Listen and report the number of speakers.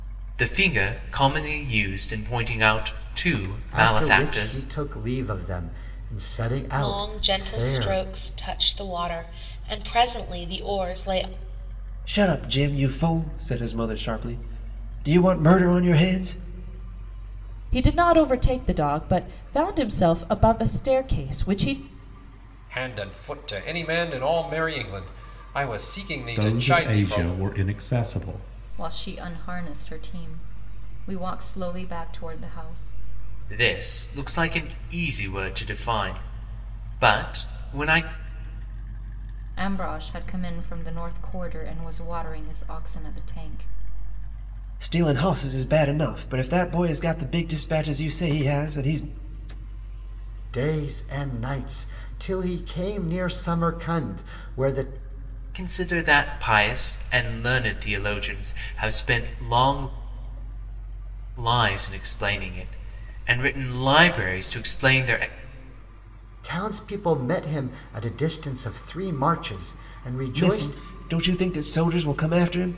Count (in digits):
8